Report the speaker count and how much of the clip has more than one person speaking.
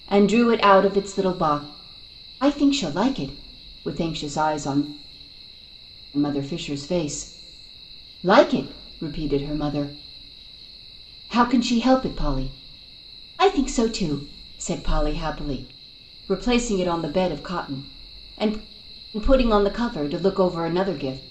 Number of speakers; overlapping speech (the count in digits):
1, no overlap